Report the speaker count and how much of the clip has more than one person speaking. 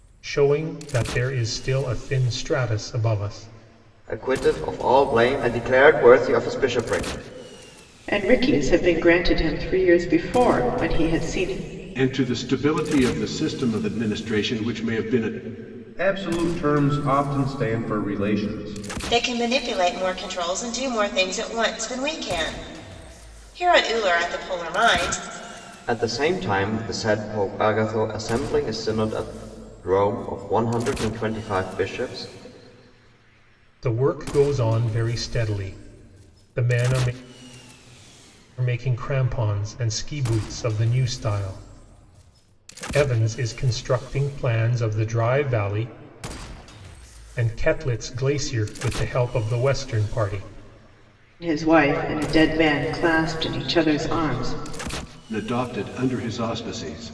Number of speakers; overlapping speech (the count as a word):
six, no overlap